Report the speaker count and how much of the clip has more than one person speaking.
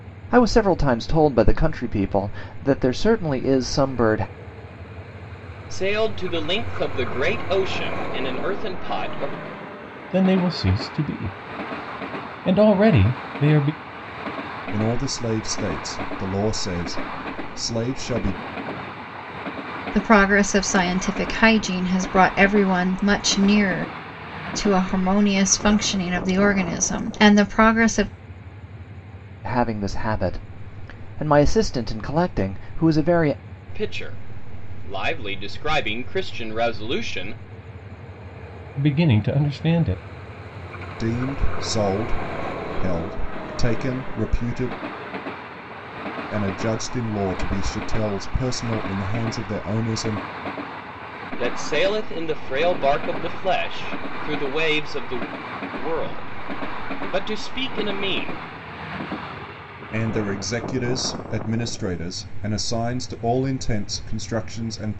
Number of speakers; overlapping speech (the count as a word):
five, no overlap